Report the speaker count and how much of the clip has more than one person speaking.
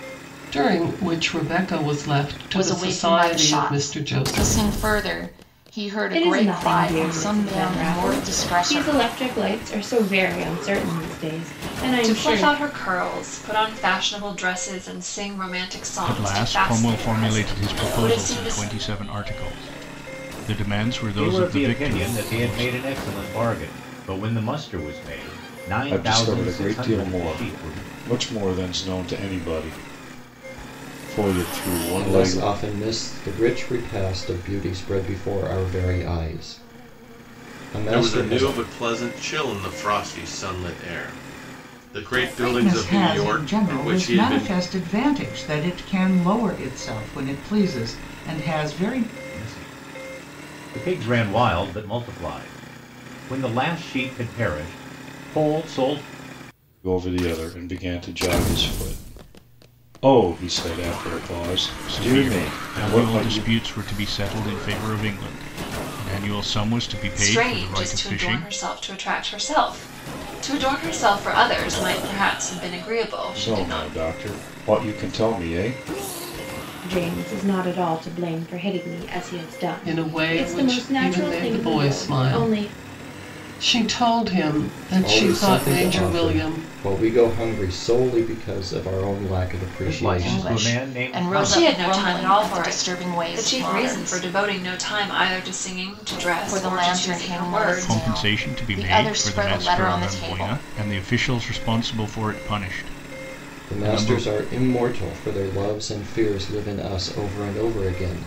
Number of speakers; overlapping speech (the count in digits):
10, about 30%